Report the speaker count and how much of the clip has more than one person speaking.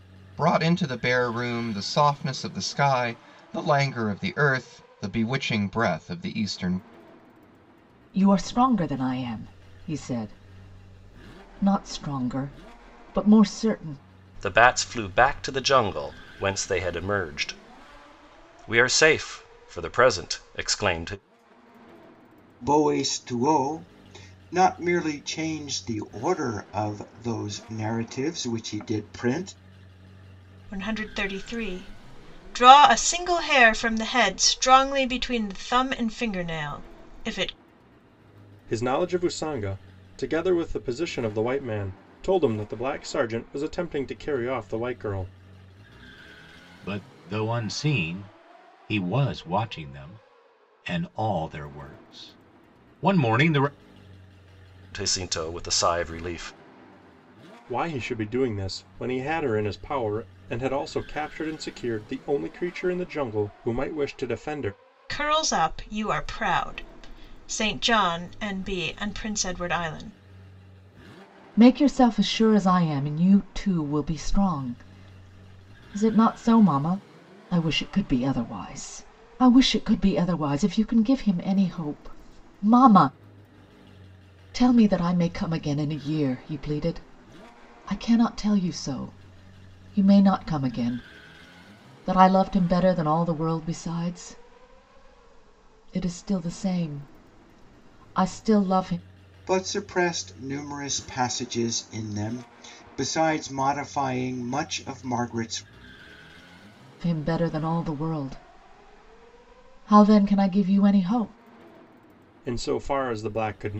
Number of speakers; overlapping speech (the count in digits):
7, no overlap